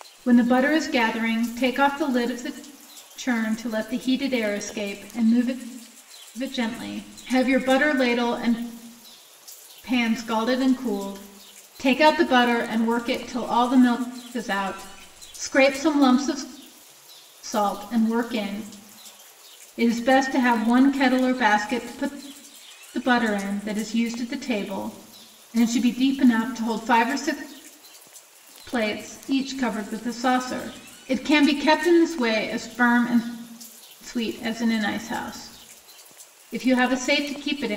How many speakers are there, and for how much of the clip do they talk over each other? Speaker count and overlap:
1, no overlap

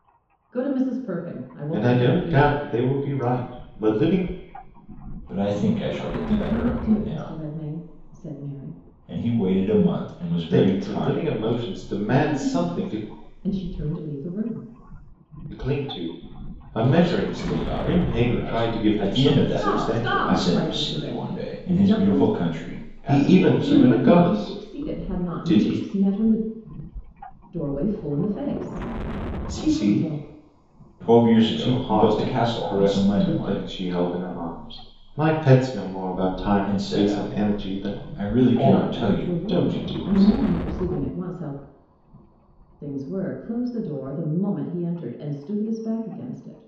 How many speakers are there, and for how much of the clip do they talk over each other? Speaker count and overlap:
3, about 41%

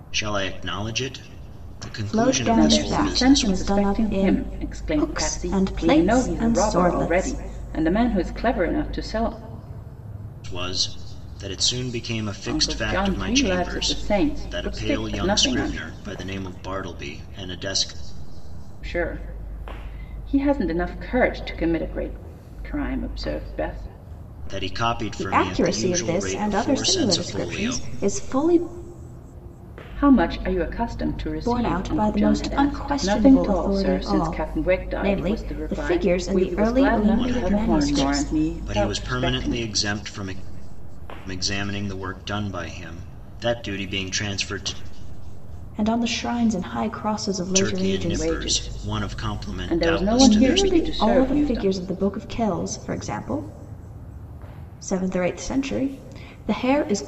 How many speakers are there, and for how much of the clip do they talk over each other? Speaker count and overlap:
3, about 39%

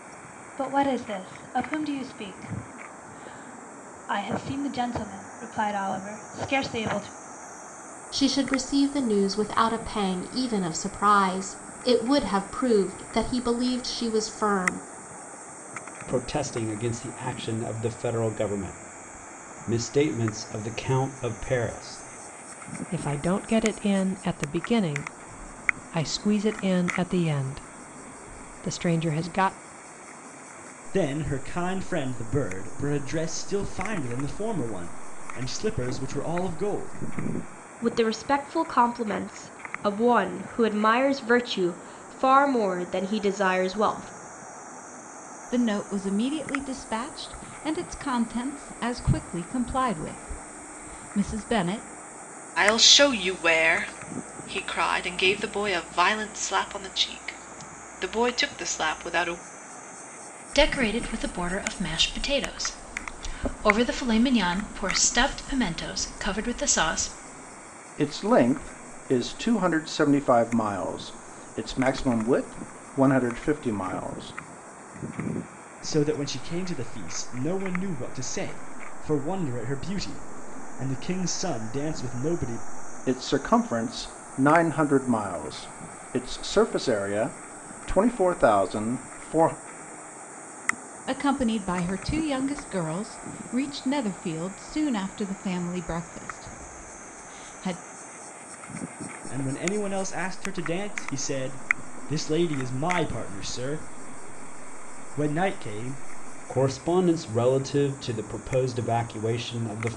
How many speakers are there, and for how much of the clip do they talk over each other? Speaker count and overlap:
10, no overlap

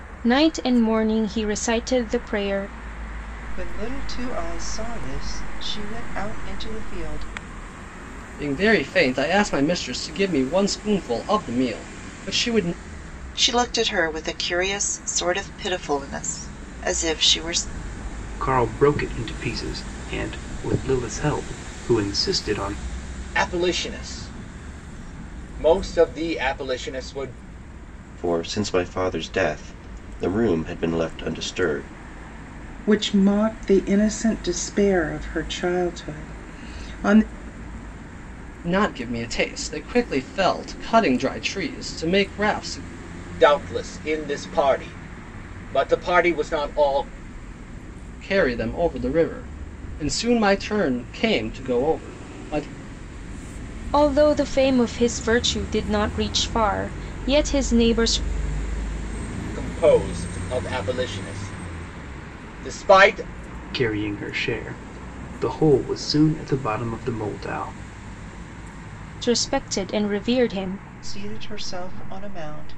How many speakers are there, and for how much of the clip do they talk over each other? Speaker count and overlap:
8, no overlap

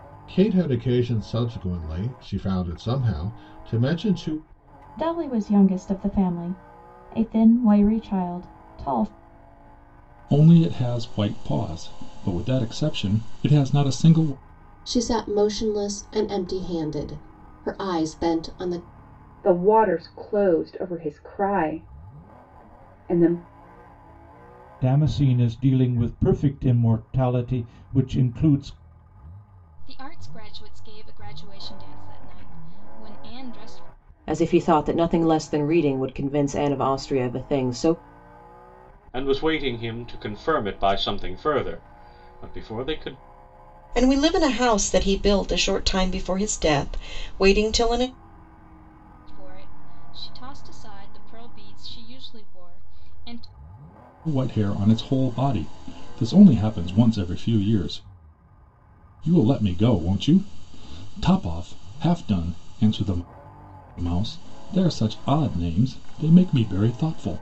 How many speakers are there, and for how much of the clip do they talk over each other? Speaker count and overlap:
10, no overlap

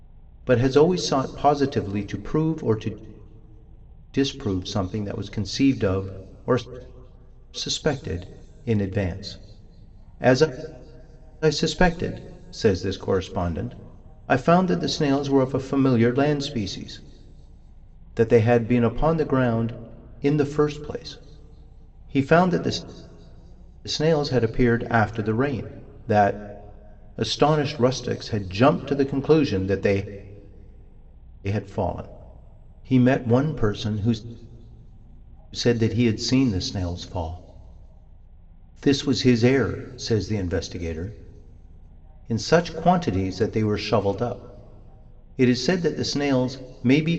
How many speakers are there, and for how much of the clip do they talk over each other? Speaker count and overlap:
1, no overlap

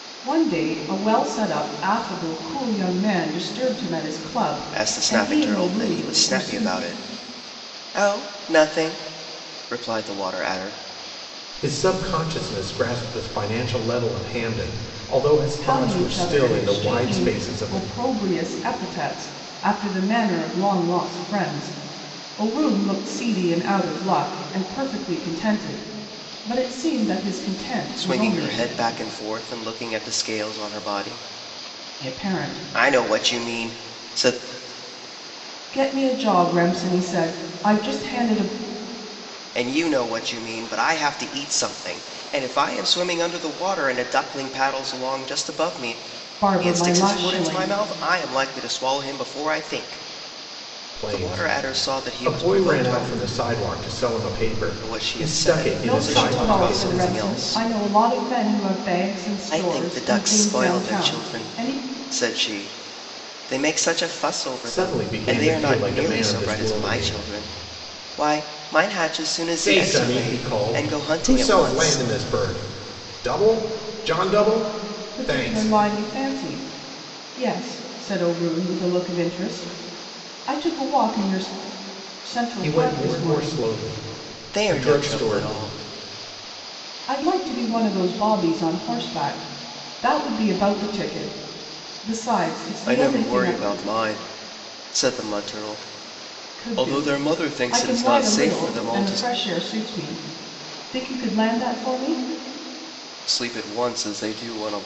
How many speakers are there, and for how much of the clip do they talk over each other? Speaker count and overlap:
3, about 26%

